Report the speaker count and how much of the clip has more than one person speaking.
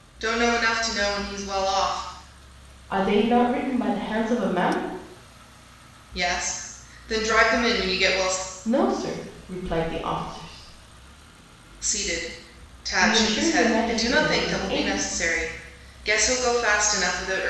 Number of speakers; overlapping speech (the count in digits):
2, about 12%